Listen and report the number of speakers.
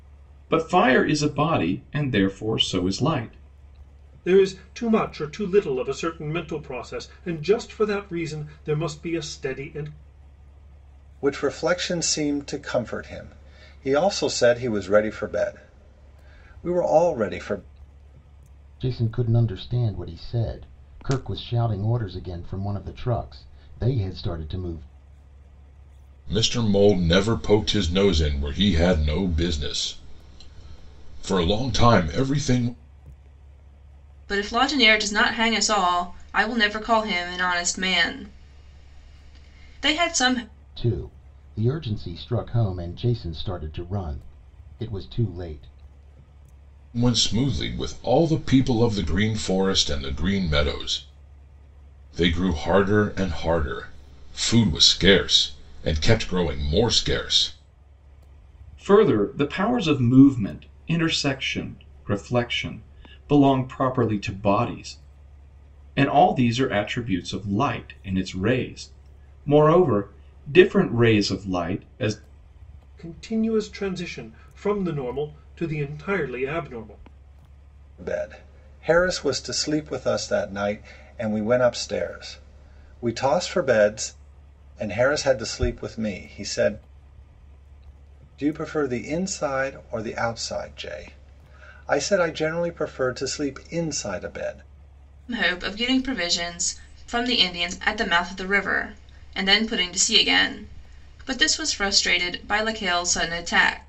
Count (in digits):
6